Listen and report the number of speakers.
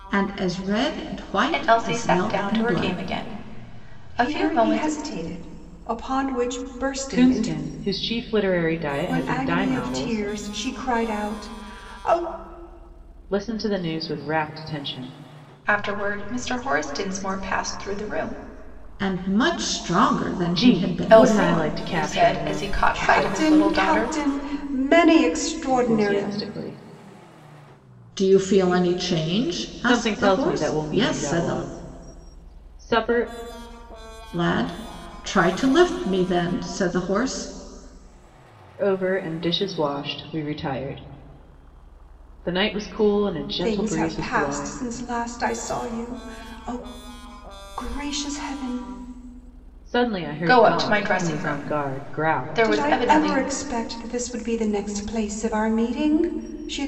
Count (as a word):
four